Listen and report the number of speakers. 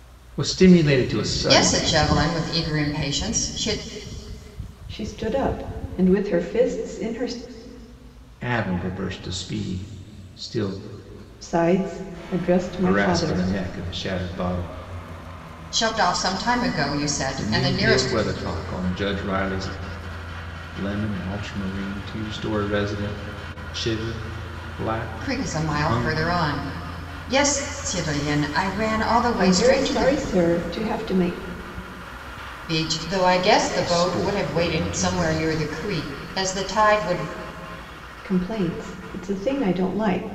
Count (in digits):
3